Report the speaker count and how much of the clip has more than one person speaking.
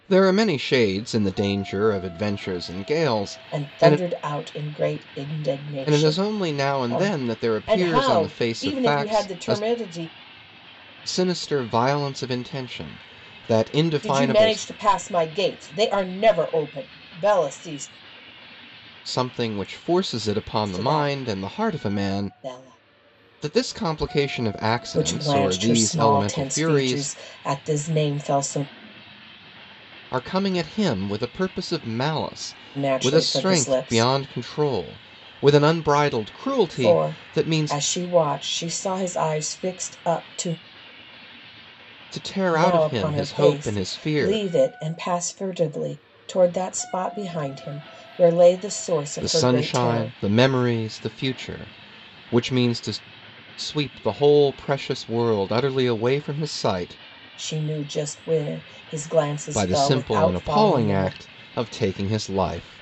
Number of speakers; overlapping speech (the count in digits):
2, about 25%